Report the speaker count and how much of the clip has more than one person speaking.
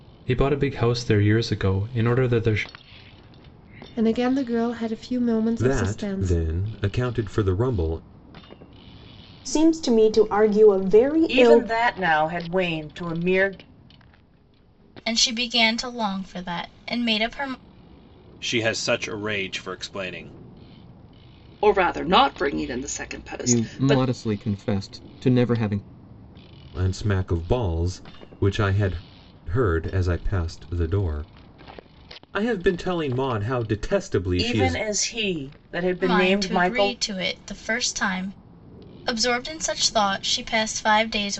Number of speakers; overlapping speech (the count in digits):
9, about 8%